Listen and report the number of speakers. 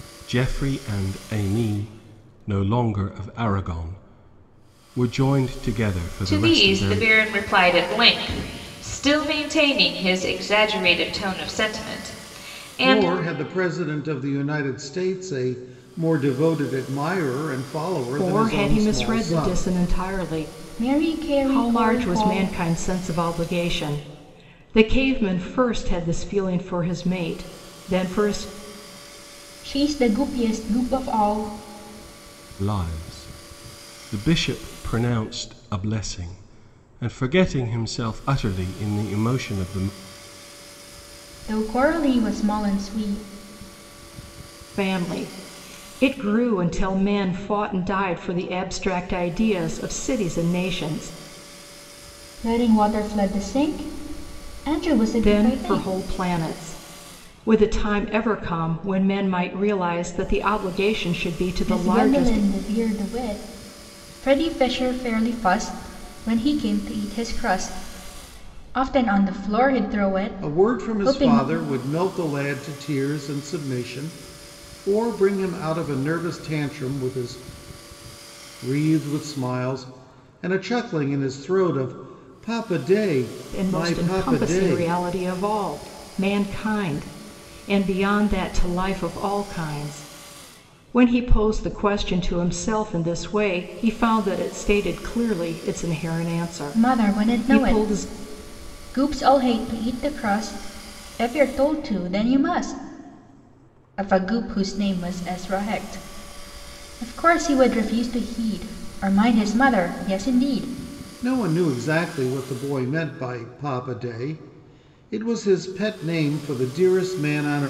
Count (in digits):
5